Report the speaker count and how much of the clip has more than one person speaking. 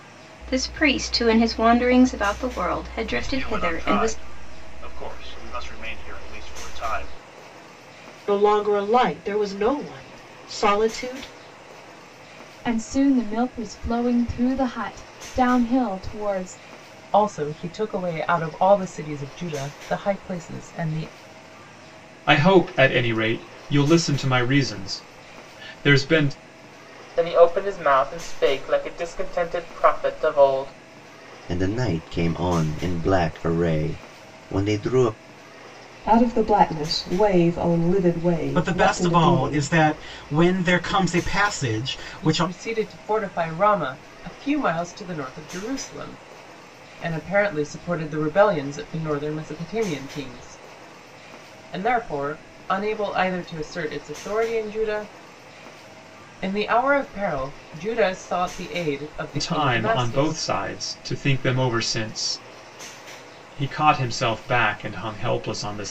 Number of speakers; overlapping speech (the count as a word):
ten, about 6%